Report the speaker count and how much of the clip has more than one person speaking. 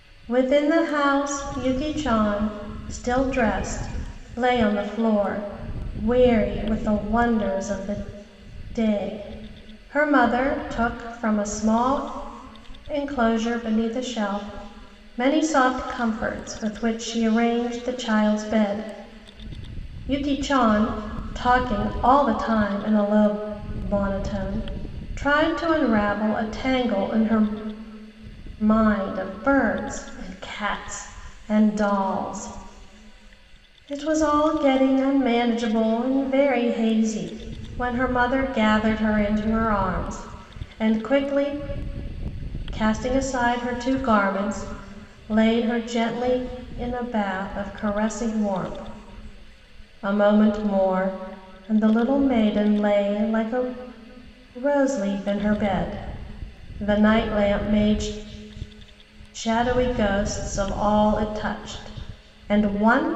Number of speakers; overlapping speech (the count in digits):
1, no overlap